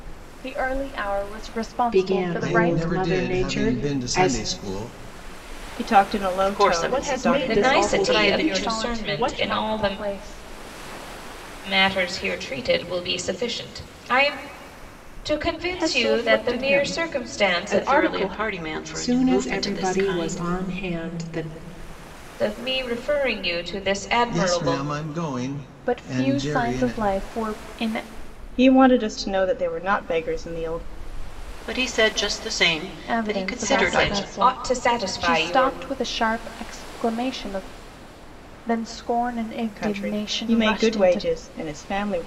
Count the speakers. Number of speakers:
7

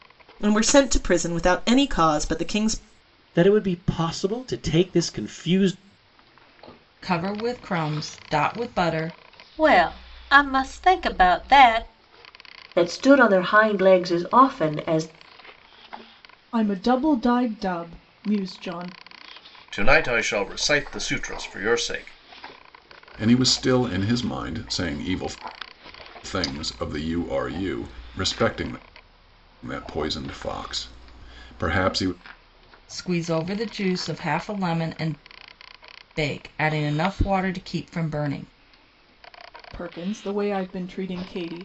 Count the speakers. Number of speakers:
8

